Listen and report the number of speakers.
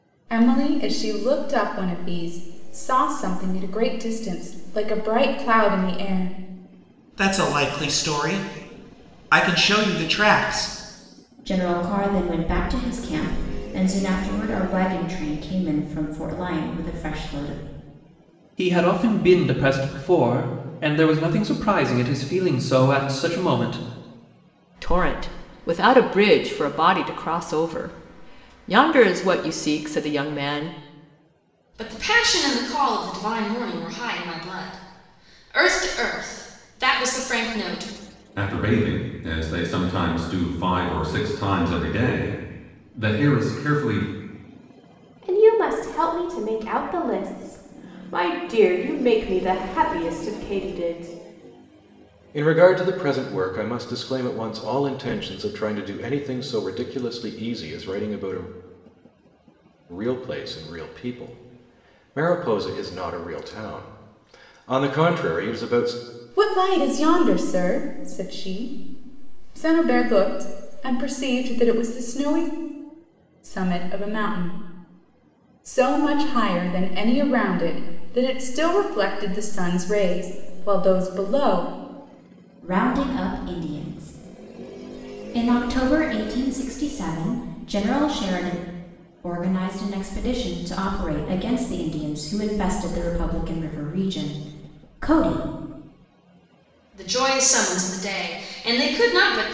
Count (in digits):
9